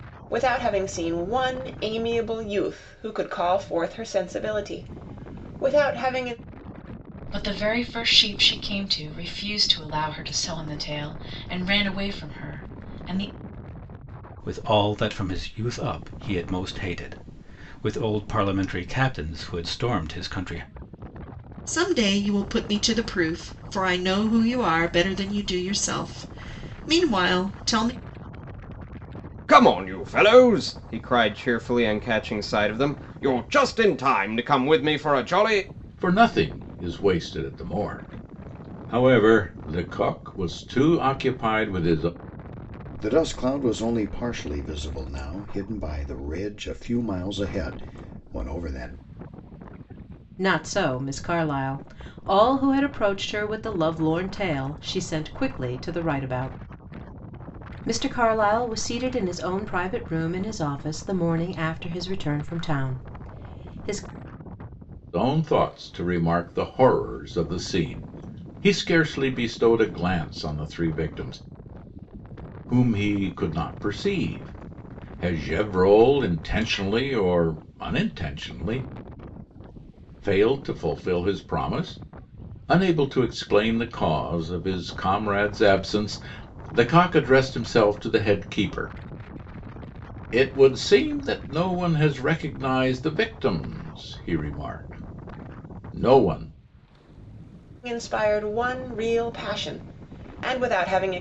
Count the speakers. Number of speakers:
8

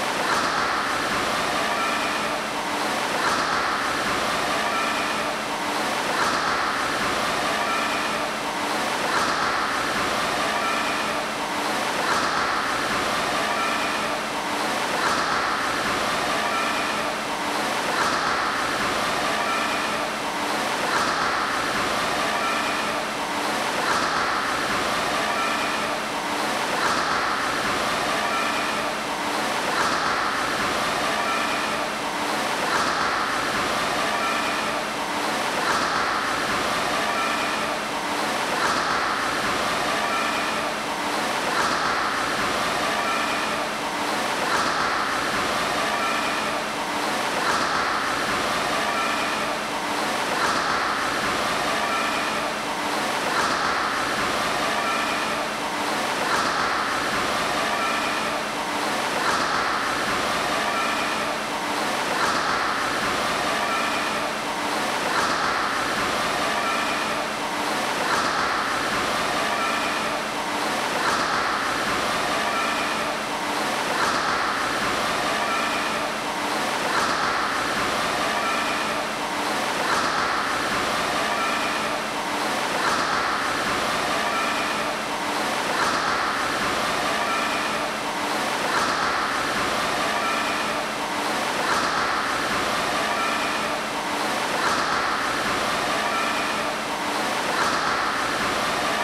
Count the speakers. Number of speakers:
0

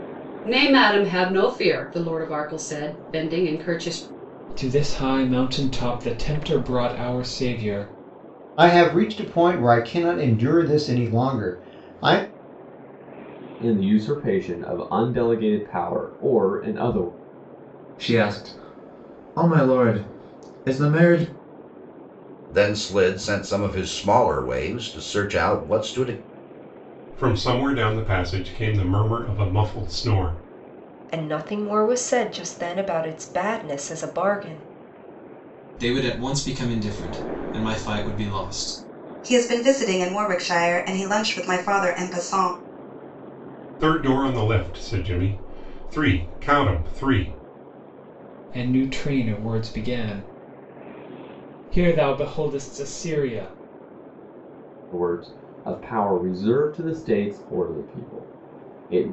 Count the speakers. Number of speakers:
10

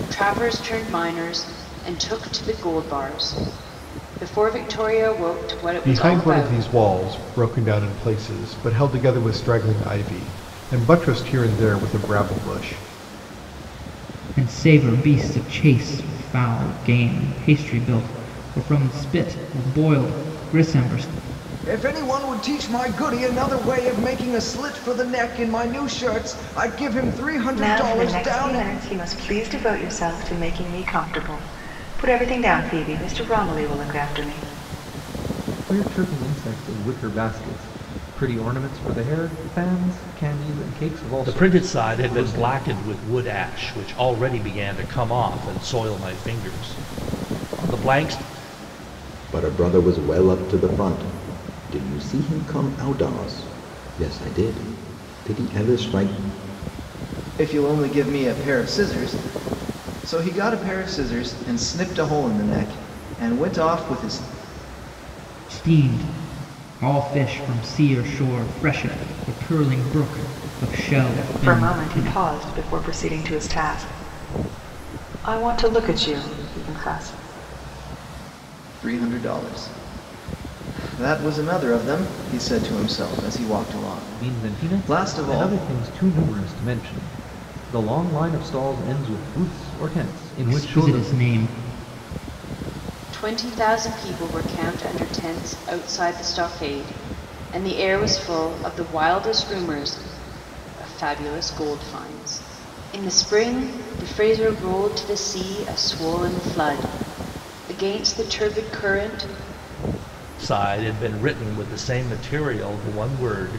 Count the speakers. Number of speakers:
8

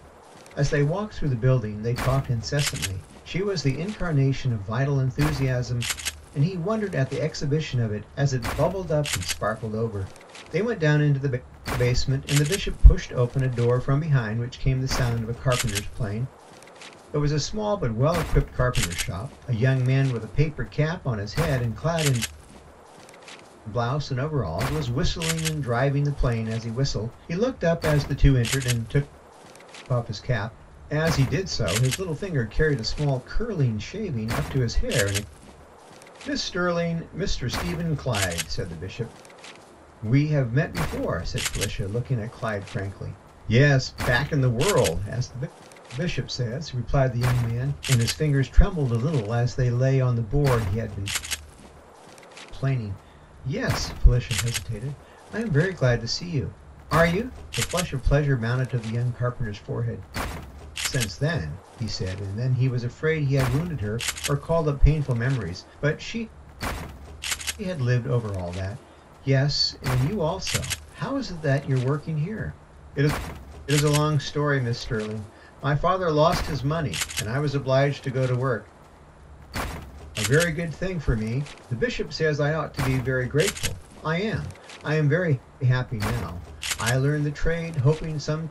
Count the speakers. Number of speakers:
1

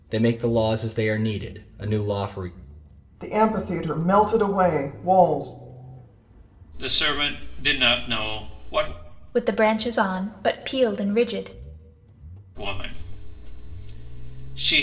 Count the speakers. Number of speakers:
4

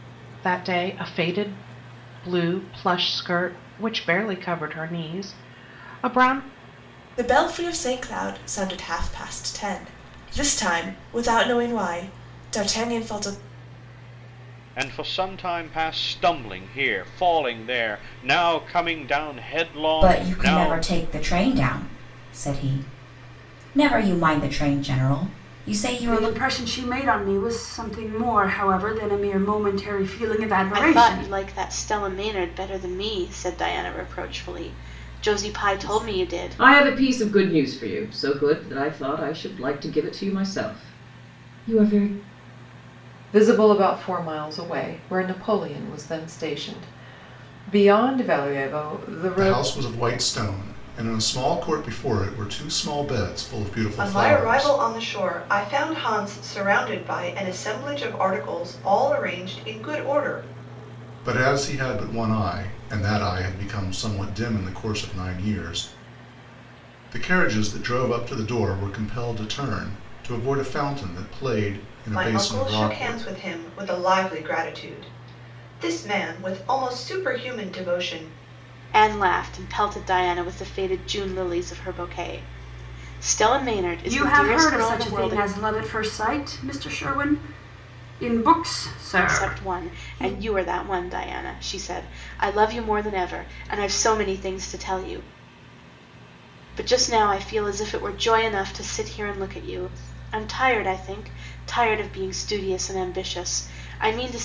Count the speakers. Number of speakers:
10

